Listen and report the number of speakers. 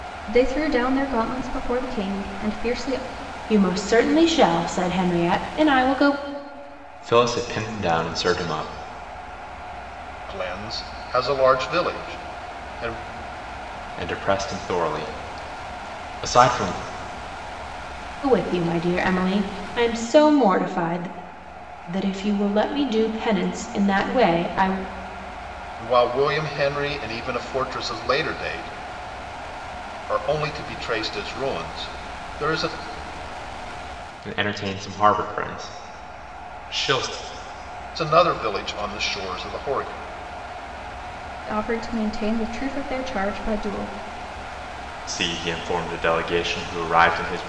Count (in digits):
4